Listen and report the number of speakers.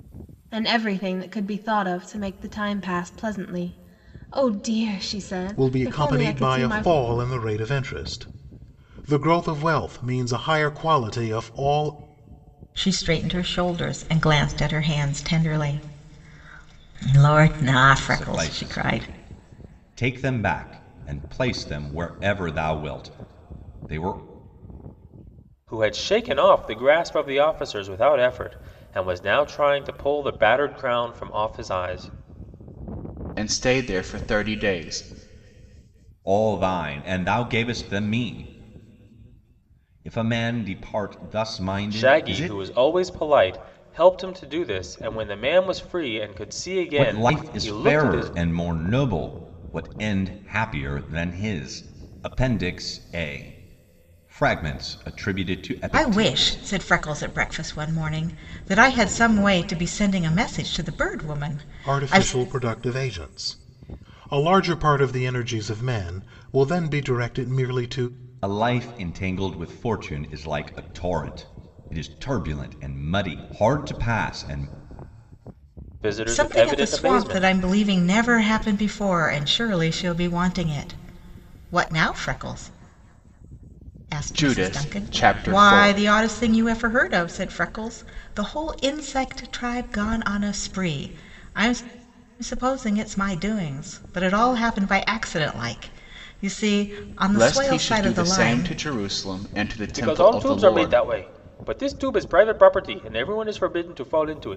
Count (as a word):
six